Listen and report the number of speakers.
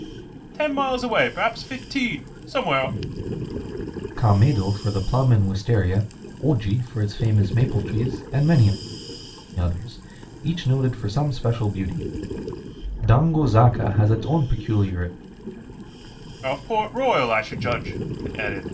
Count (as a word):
two